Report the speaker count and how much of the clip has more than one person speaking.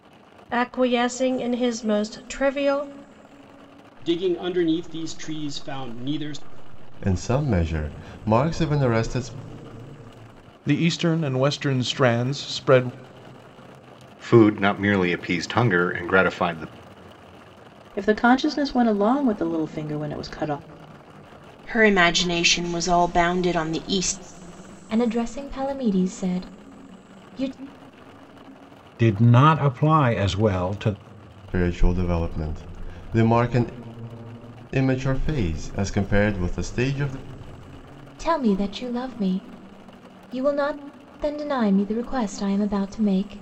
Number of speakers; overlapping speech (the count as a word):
nine, no overlap